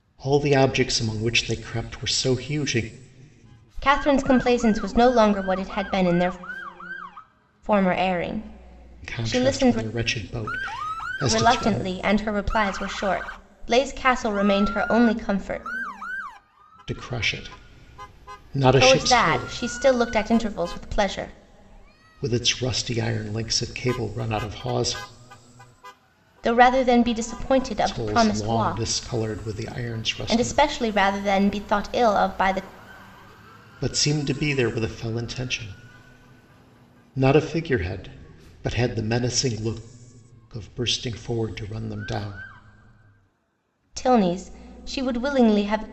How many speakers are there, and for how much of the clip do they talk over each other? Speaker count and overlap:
two, about 8%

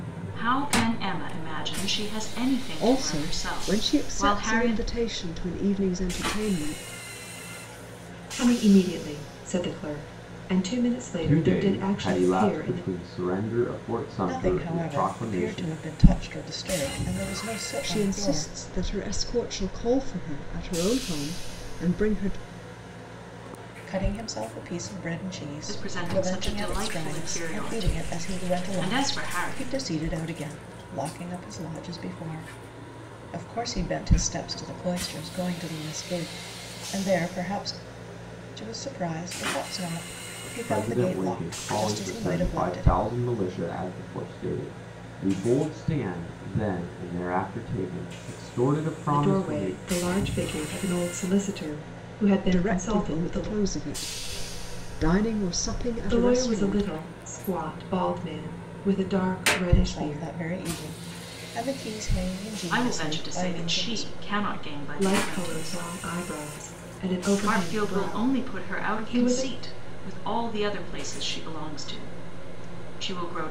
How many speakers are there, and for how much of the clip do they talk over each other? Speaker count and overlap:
five, about 28%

